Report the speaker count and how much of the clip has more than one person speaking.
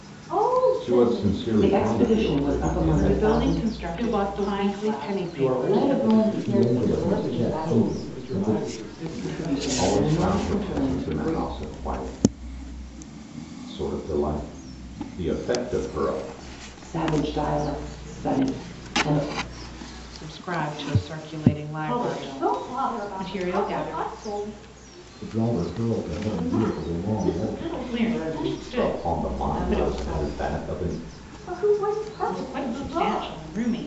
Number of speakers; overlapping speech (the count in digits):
8, about 53%